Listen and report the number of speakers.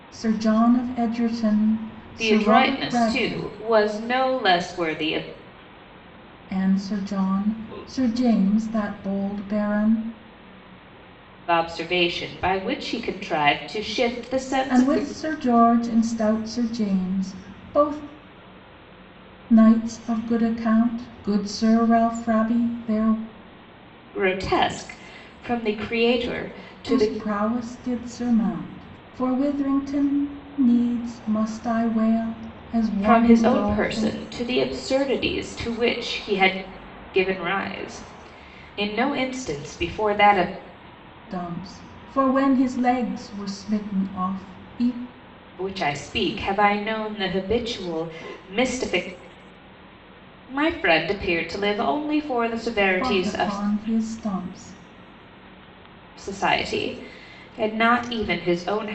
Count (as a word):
two